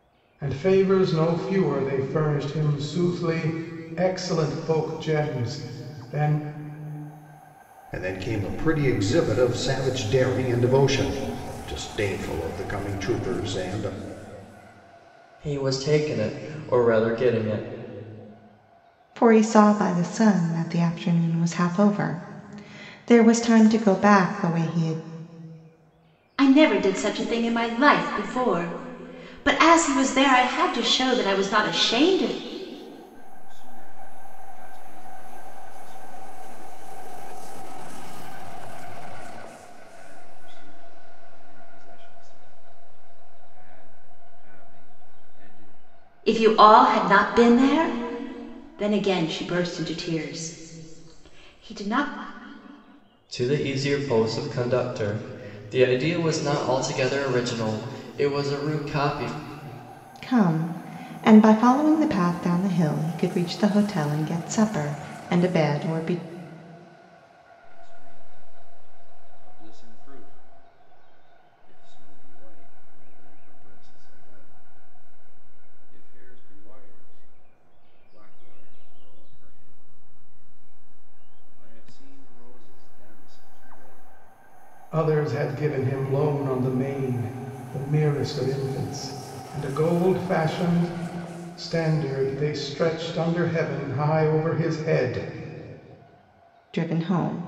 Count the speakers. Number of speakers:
six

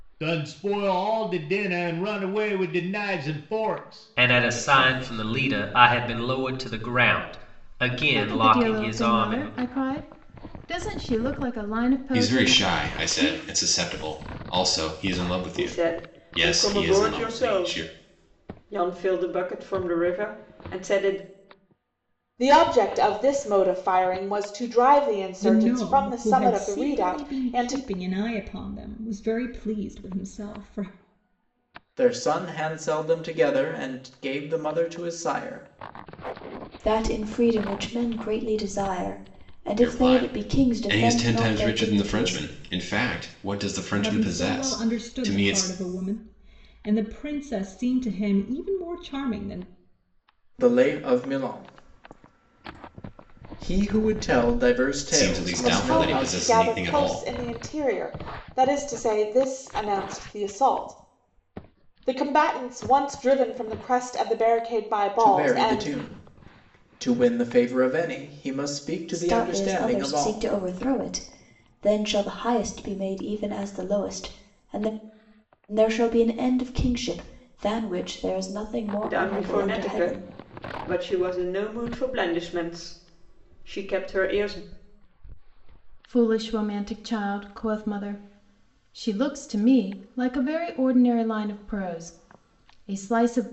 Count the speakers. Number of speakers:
nine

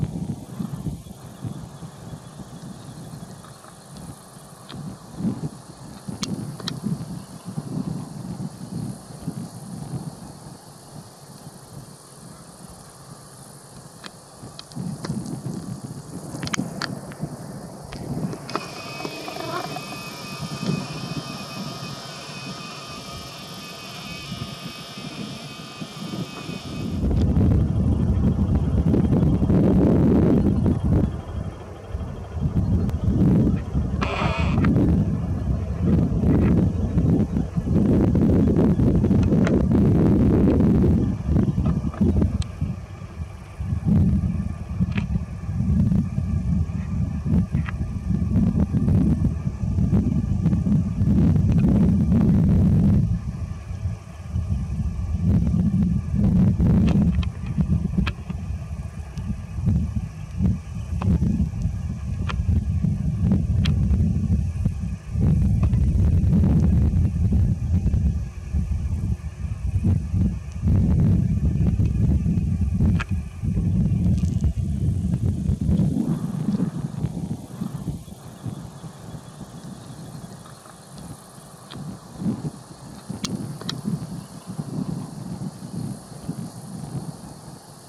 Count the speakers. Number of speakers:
zero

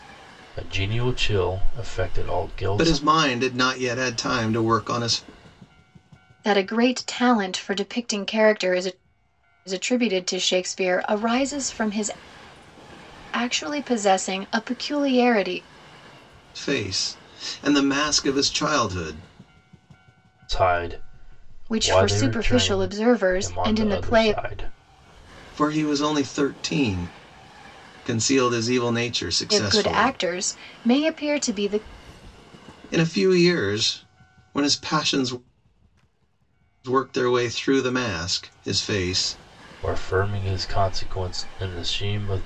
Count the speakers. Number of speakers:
three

